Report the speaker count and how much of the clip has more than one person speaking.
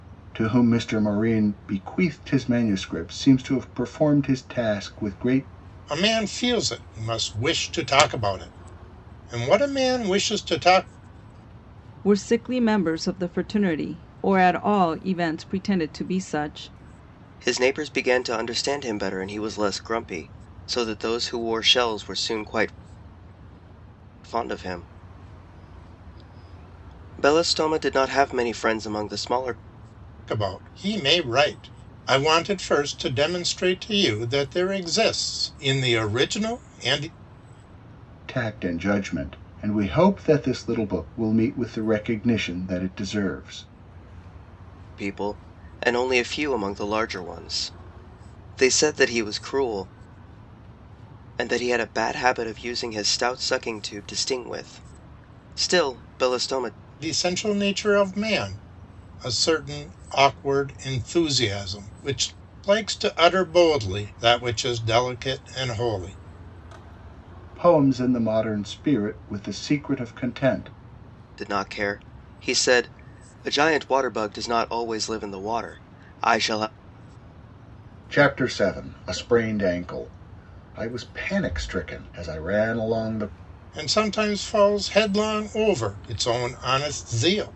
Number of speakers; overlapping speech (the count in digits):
4, no overlap